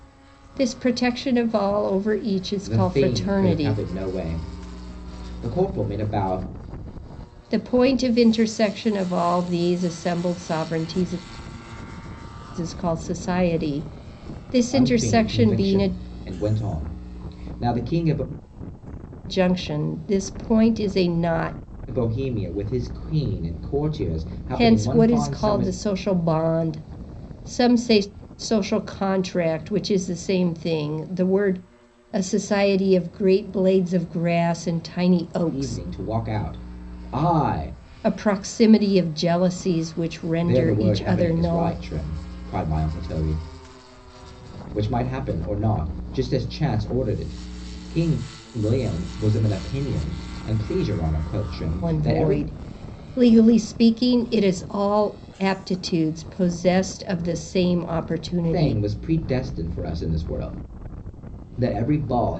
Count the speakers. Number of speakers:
2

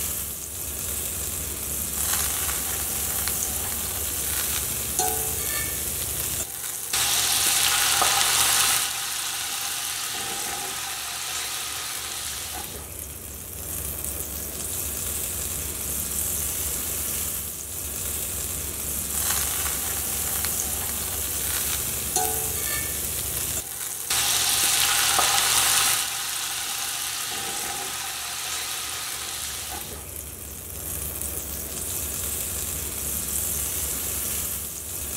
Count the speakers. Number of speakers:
0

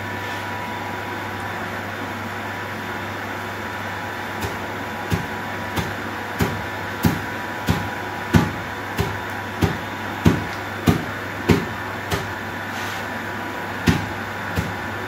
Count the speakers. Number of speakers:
0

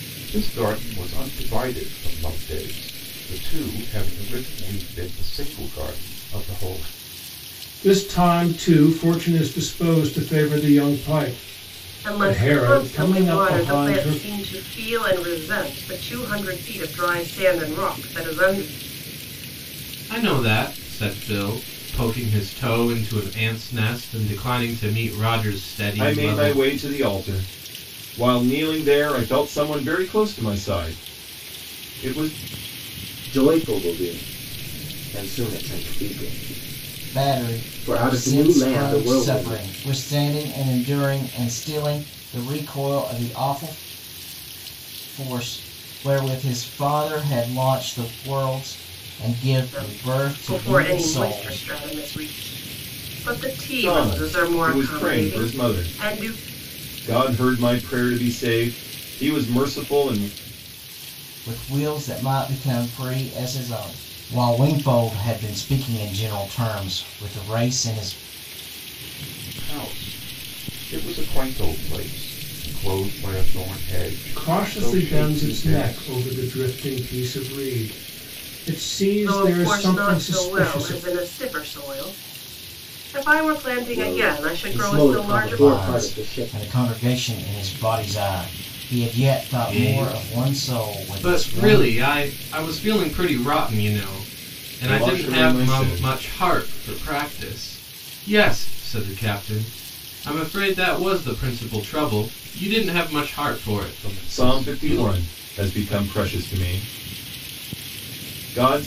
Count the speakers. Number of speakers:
7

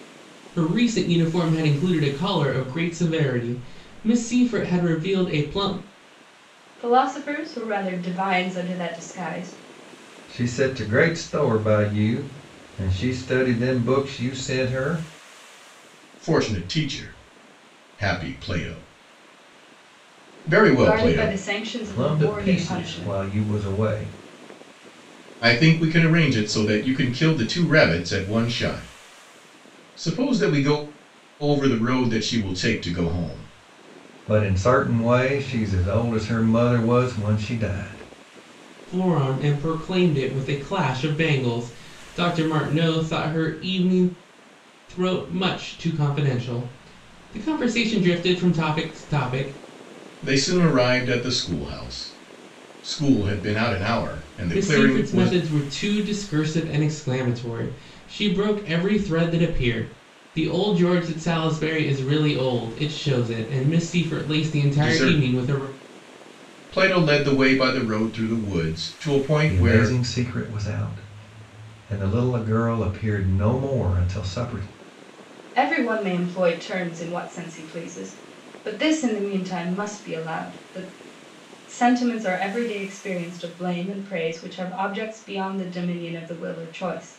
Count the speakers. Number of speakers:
4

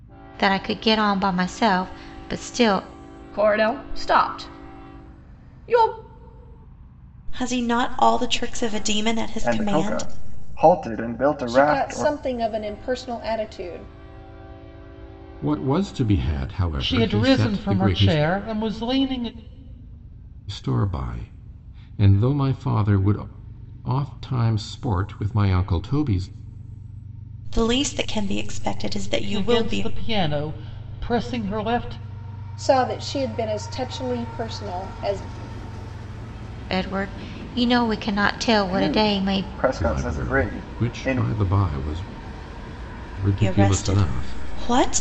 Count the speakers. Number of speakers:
7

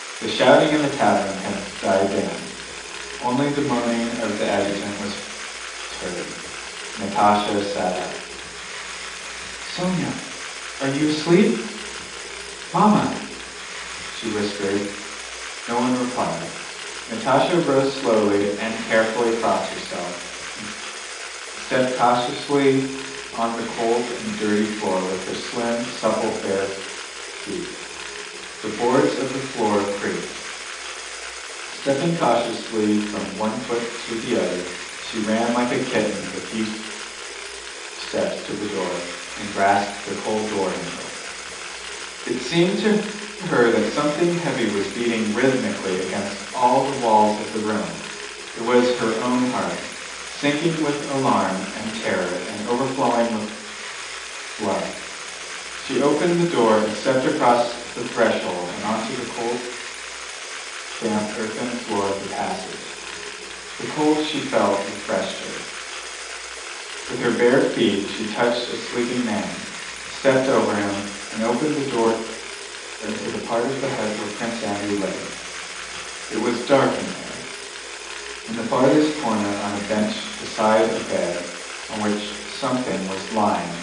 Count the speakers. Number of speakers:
1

